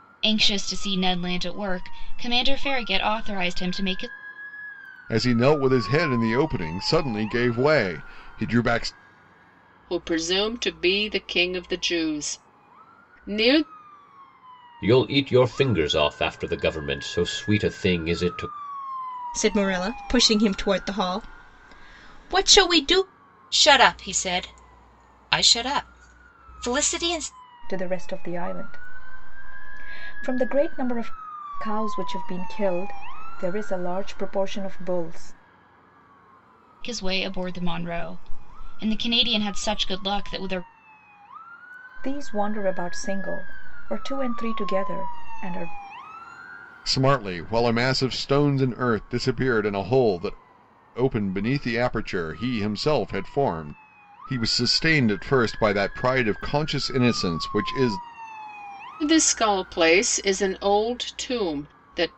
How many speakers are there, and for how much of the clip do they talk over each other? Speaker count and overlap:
seven, no overlap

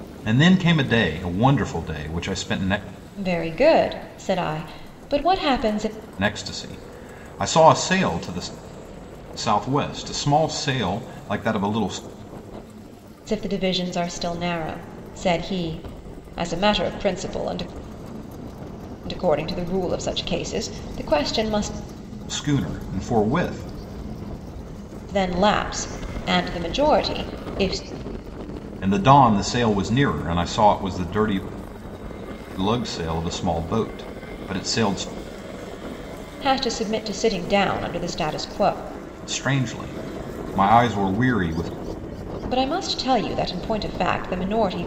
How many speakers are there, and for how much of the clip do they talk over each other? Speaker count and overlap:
two, no overlap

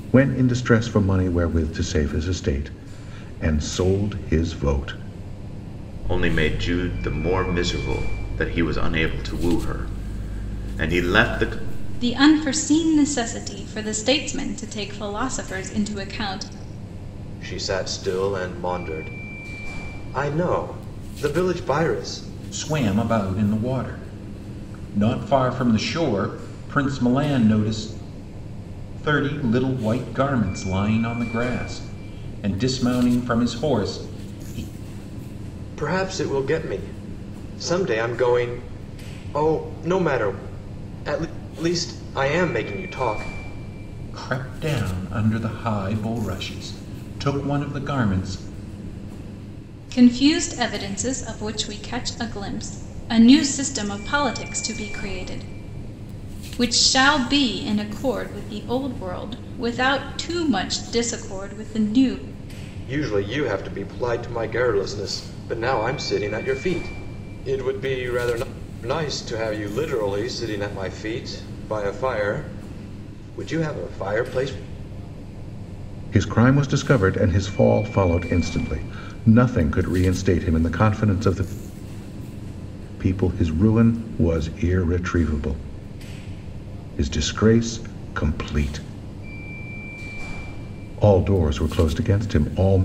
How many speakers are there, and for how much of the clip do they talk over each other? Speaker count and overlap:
five, no overlap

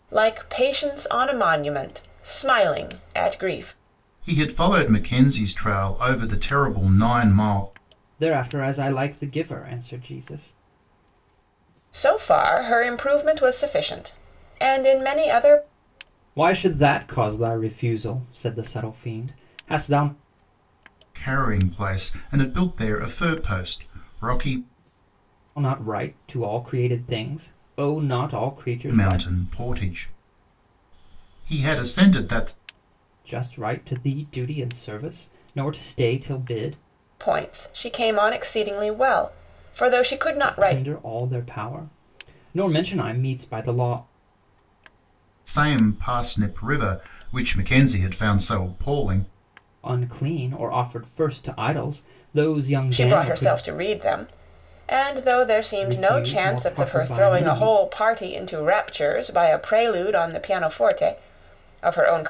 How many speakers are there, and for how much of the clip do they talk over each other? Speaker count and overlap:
three, about 6%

